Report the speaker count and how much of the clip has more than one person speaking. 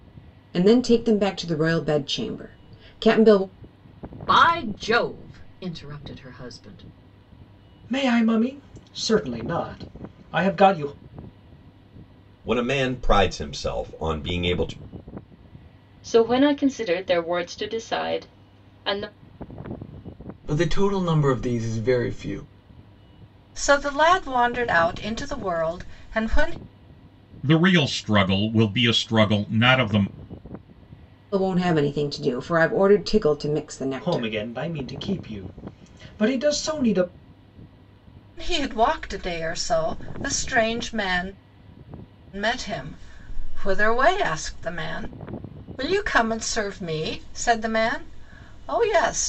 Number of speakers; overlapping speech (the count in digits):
8, about 1%